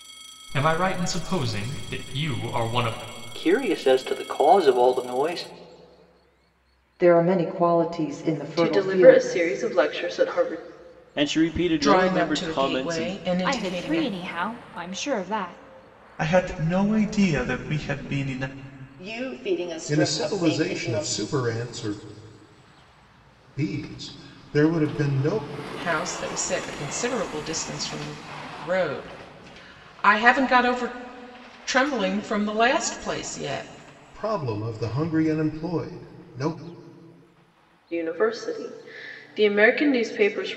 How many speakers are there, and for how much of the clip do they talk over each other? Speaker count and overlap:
10, about 10%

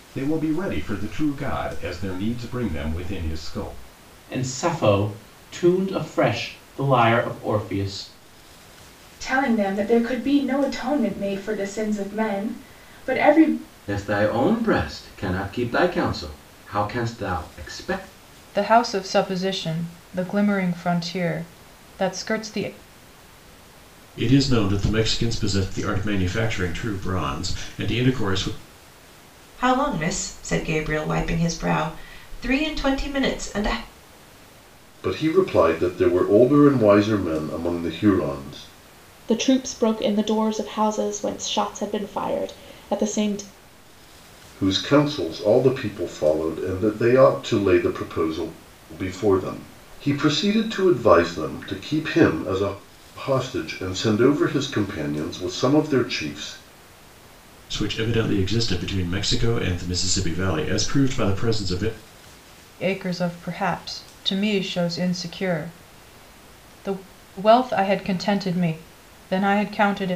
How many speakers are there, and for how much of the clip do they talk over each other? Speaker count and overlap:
9, no overlap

